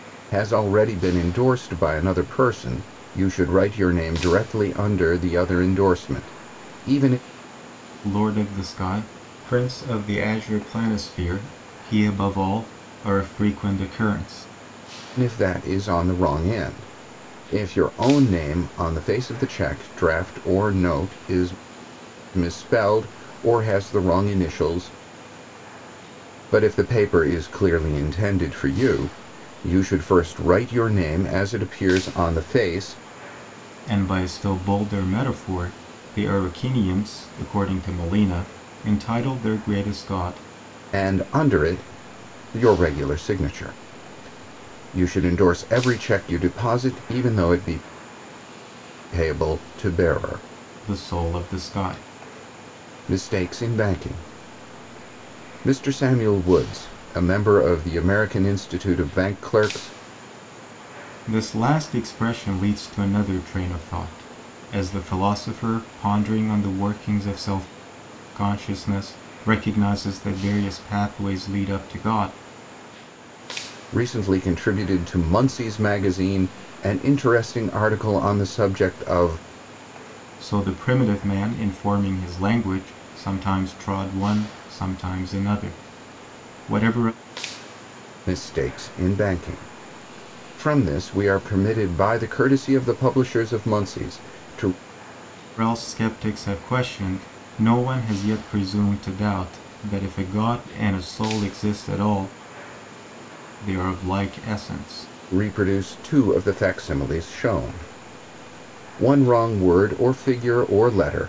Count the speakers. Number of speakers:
2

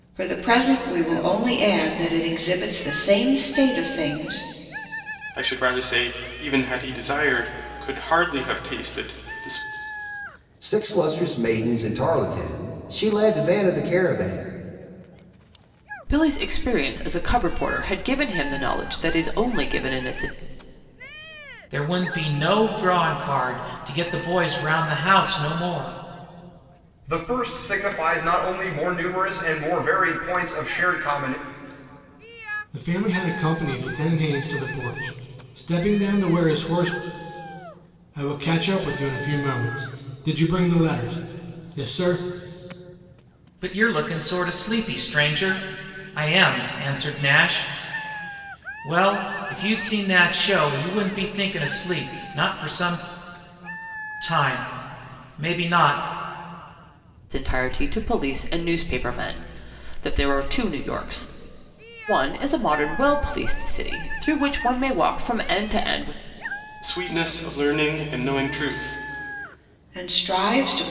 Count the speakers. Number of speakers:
7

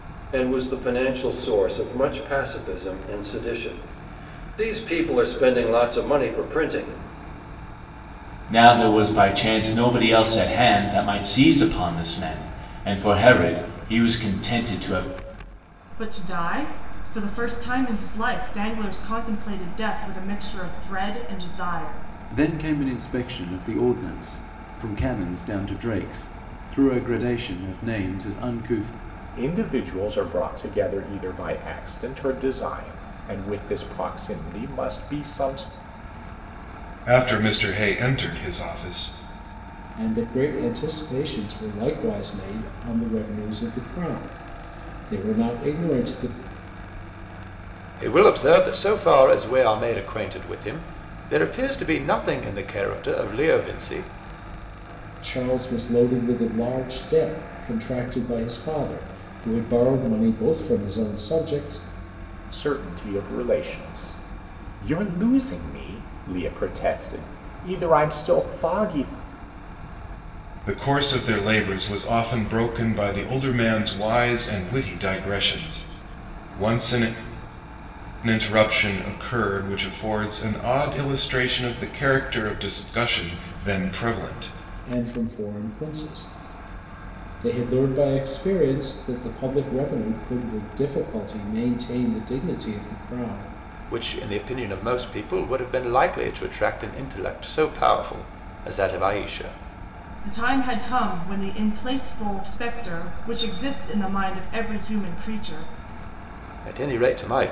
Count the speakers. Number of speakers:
8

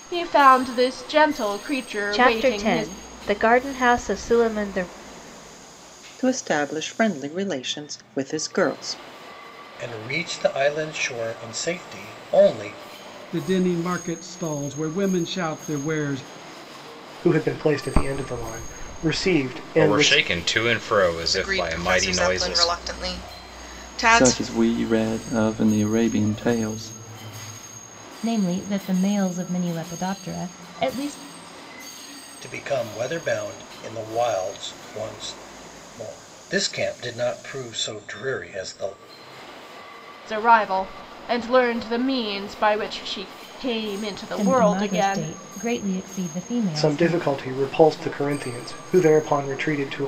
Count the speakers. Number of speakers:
10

